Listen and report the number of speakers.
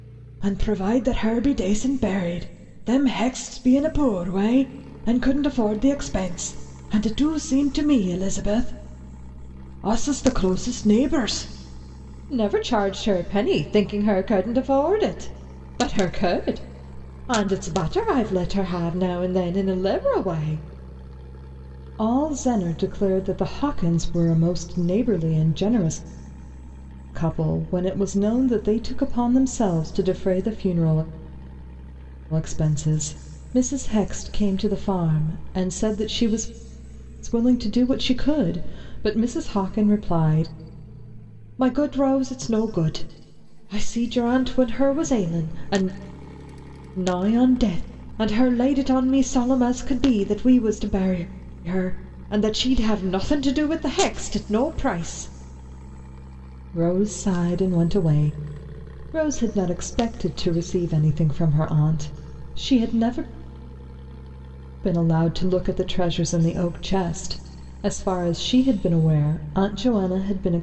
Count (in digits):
1